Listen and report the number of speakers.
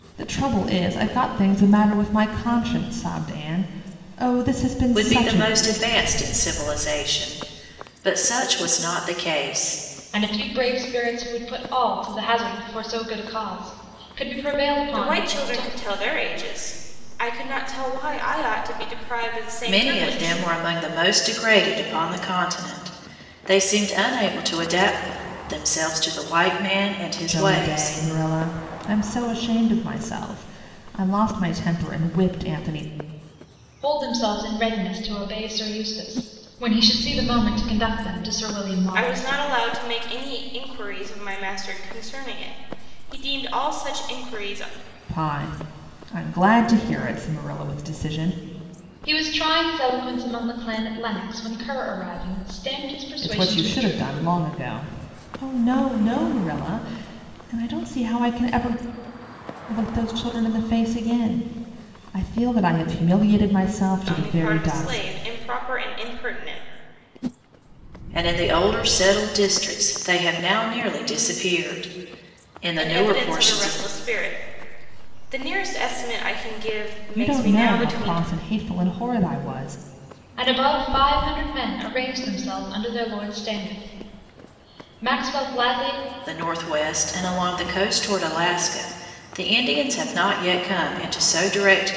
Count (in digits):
4